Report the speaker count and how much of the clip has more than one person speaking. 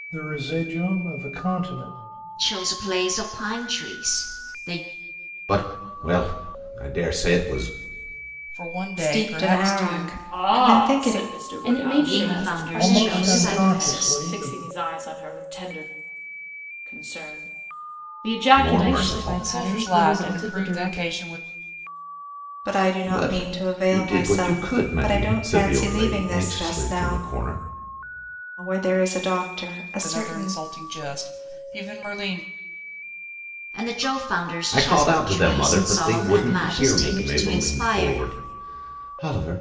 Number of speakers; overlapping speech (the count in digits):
7, about 40%